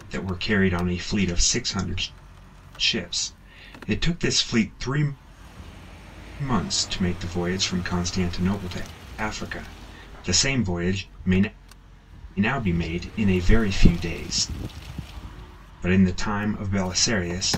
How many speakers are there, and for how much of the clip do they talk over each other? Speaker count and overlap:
1, no overlap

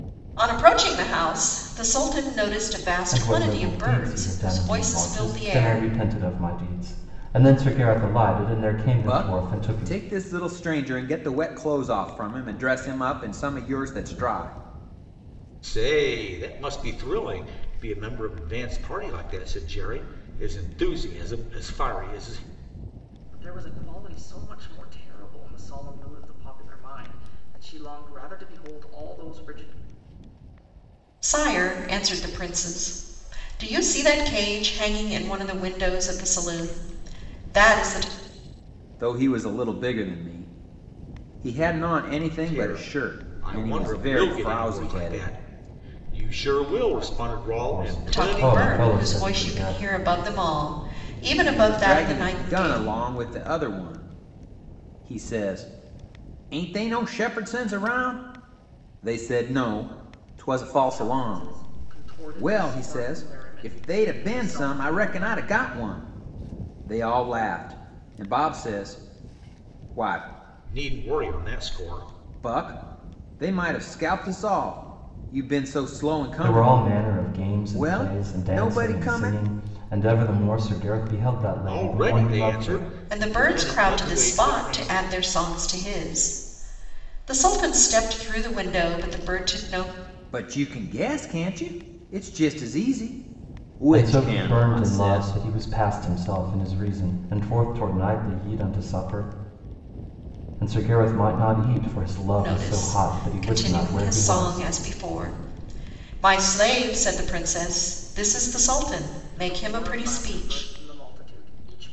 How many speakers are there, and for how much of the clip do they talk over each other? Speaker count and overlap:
5, about 23%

